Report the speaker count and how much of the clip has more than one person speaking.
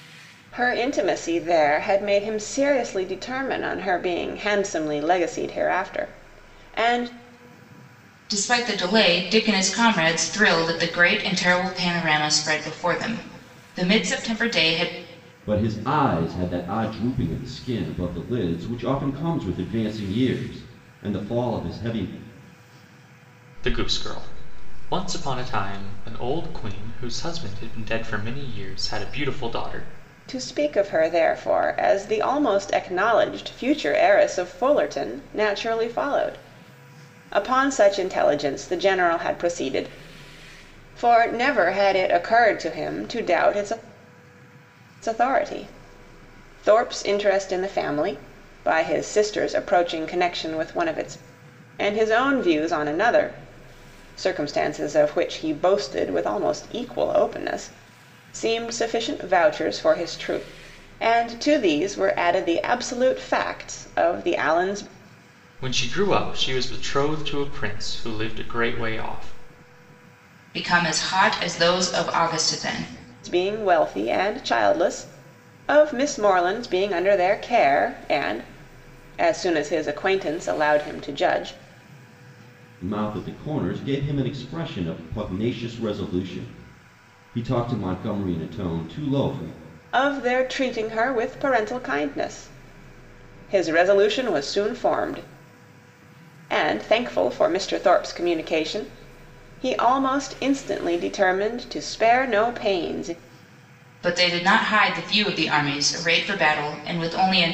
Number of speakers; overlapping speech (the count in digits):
4, no overlap